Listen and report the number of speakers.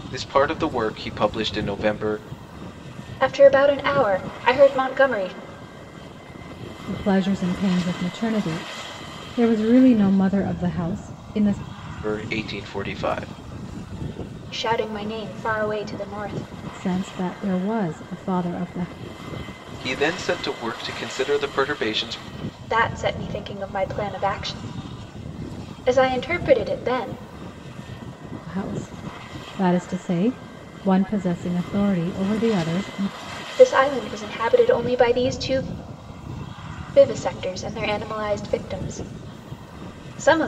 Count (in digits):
3